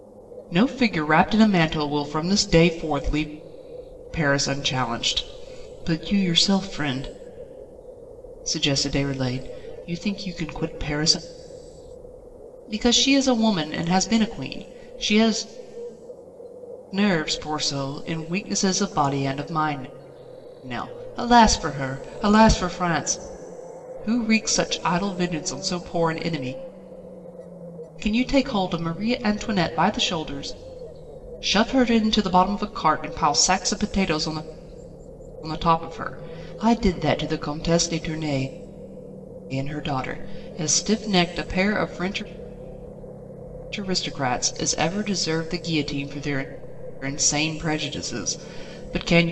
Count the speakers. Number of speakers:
1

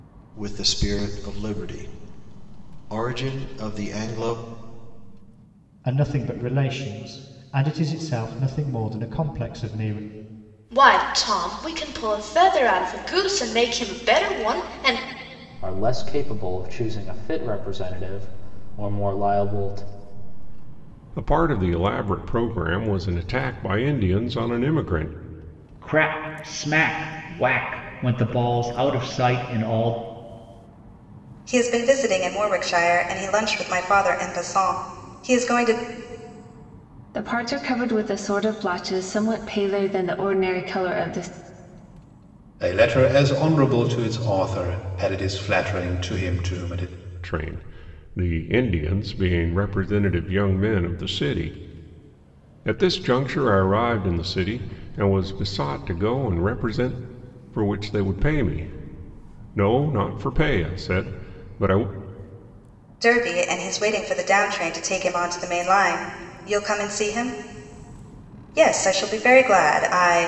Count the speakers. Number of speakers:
9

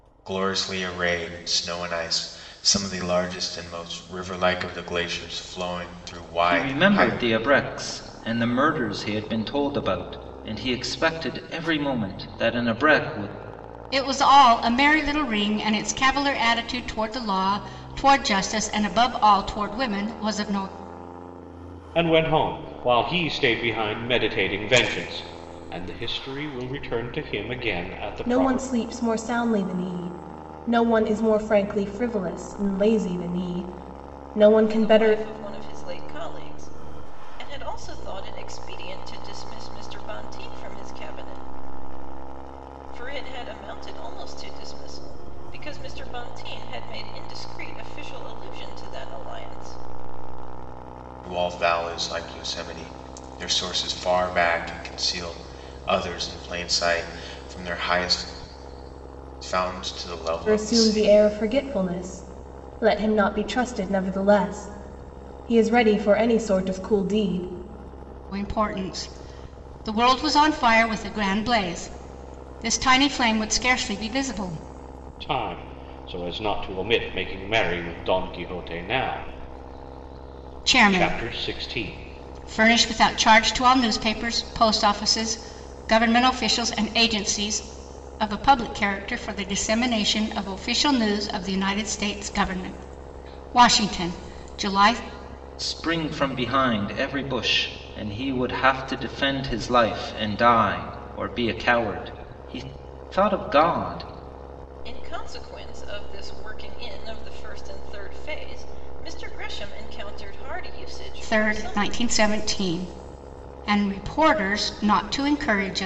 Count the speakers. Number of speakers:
6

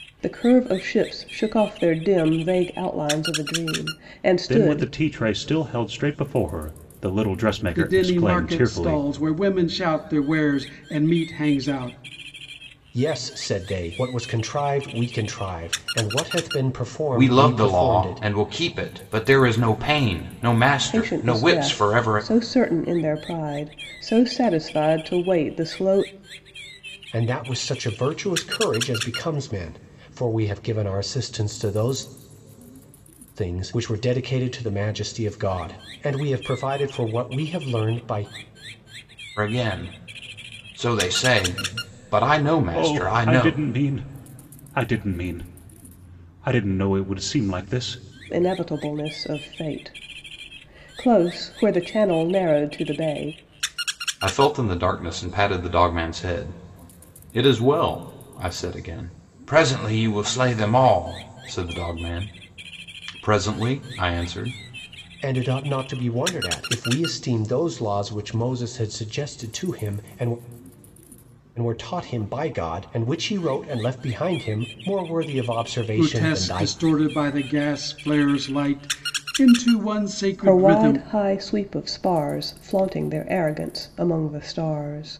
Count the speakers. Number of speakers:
5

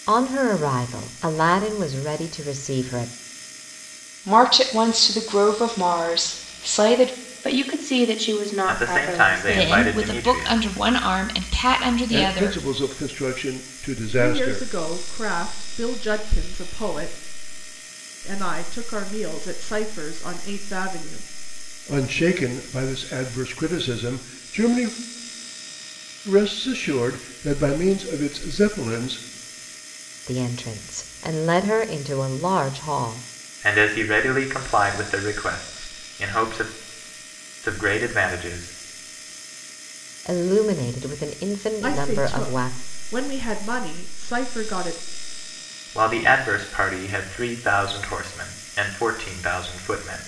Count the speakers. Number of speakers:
7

